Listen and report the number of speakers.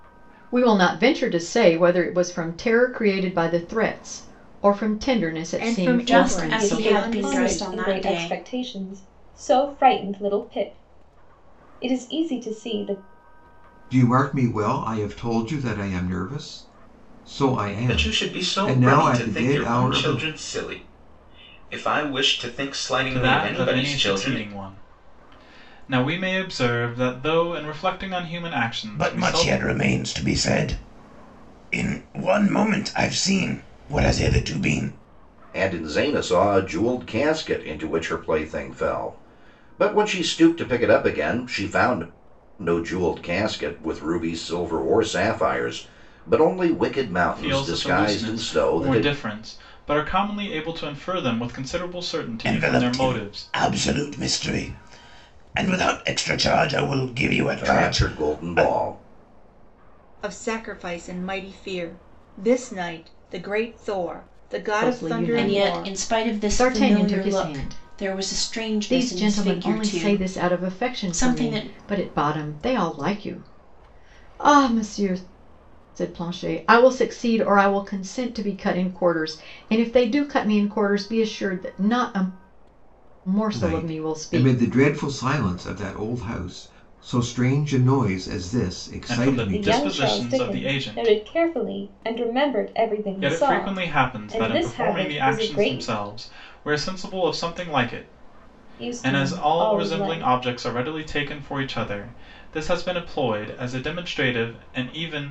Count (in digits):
9